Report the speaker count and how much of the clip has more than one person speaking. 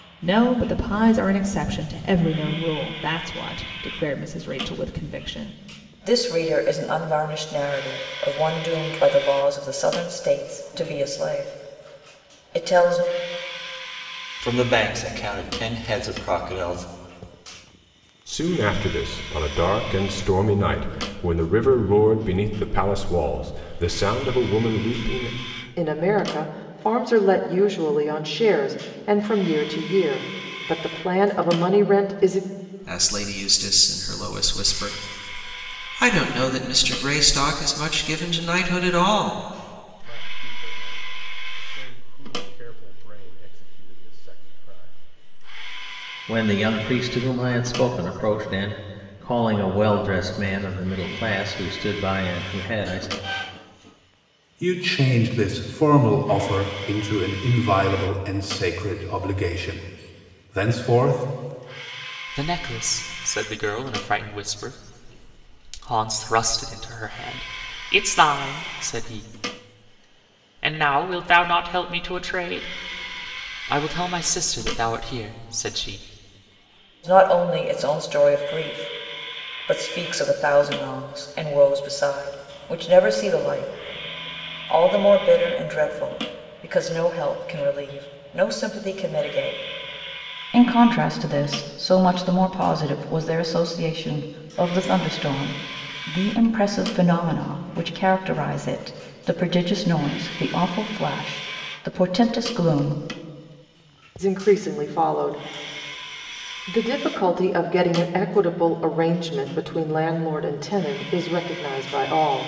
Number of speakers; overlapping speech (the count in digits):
10, no overlap